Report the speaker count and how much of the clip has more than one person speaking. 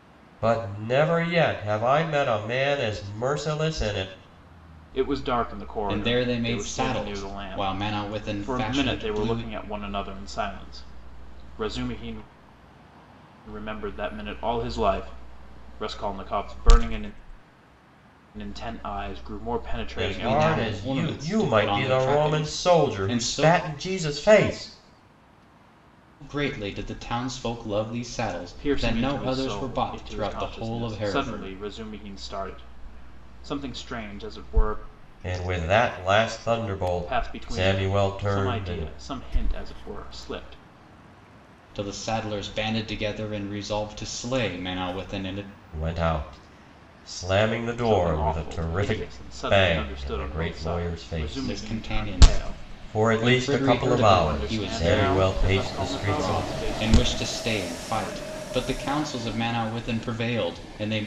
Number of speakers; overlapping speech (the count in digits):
3, about 35%